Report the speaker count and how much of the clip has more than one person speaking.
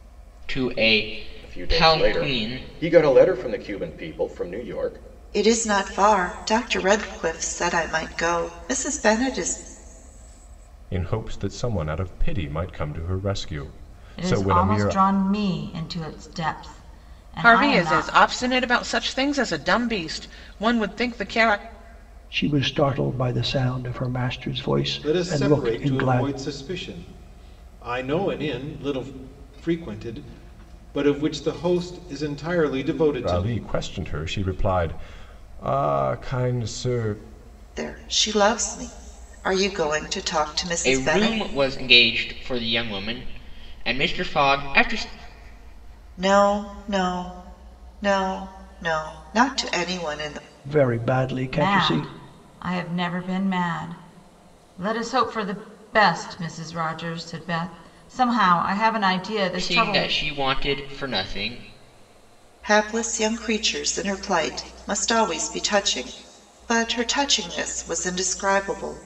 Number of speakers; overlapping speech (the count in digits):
8, about 9%